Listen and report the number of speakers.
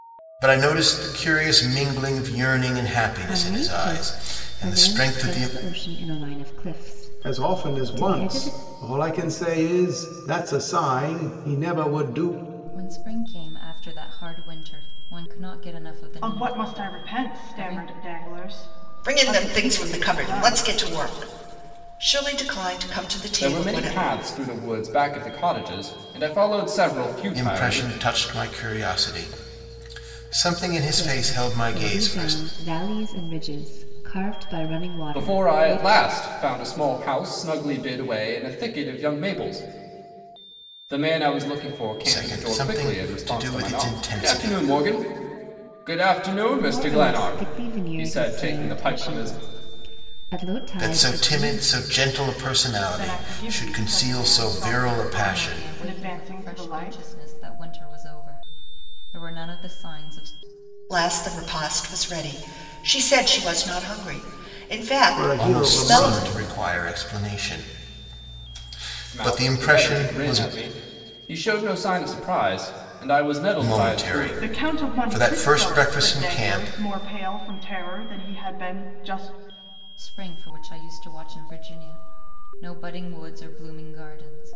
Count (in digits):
7